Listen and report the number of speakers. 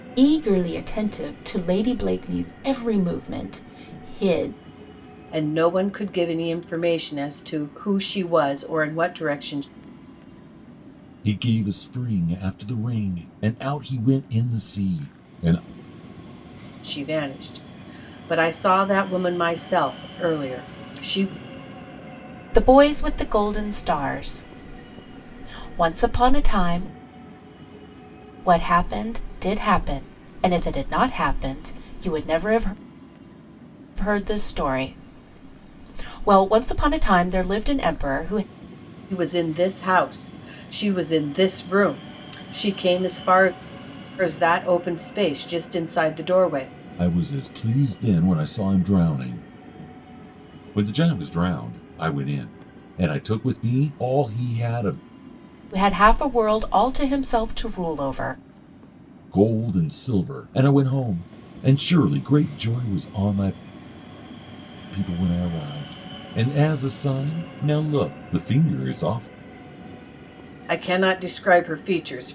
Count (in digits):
3